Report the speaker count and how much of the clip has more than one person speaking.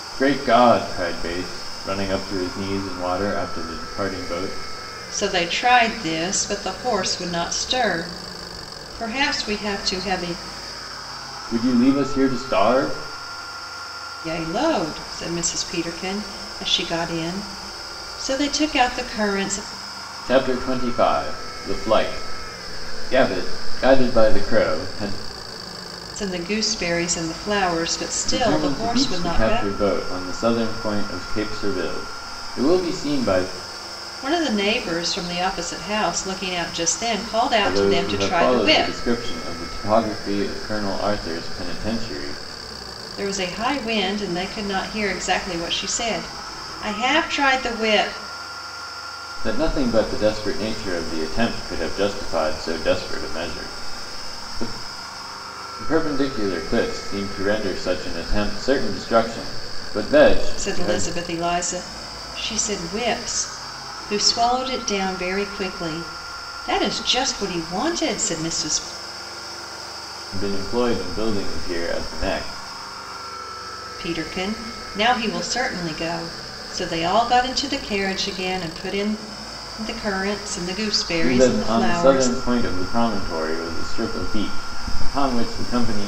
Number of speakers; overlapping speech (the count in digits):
2, about 5%